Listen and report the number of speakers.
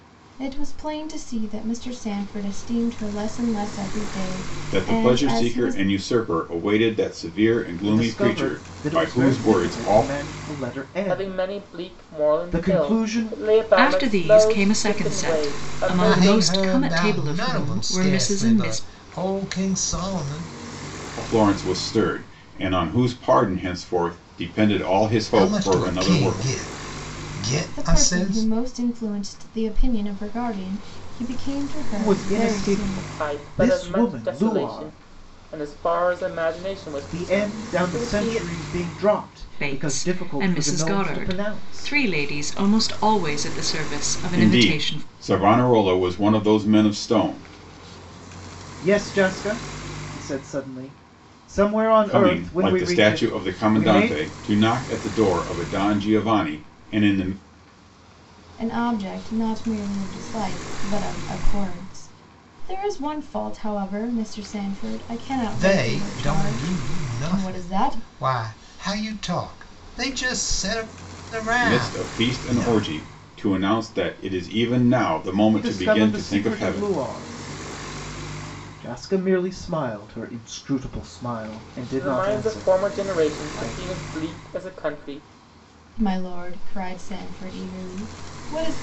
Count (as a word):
six